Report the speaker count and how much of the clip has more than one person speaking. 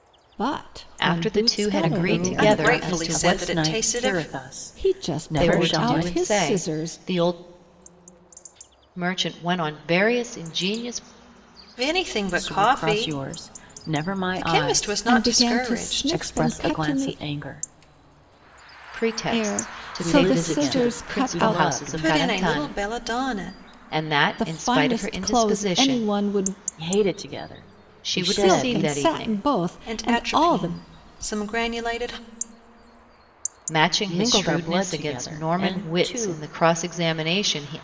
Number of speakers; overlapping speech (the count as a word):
four, about 50%